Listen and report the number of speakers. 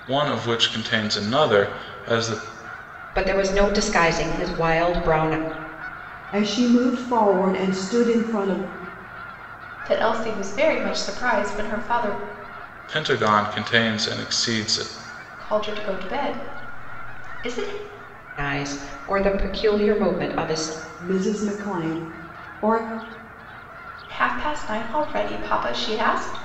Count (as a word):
four